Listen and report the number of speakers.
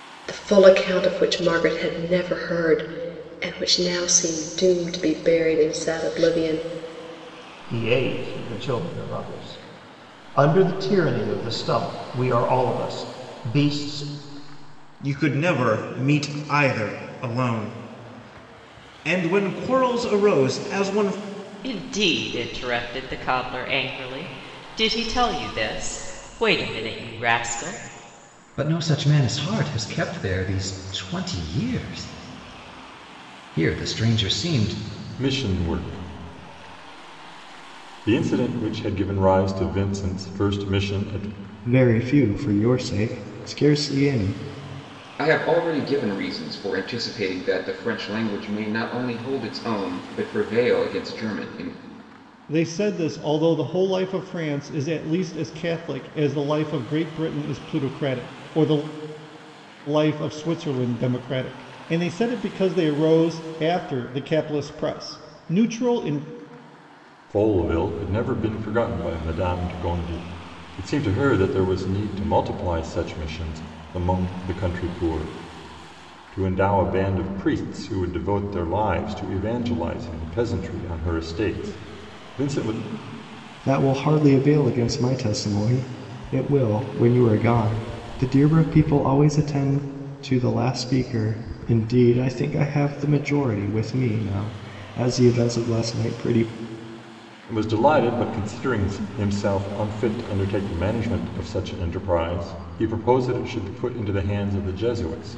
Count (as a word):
nine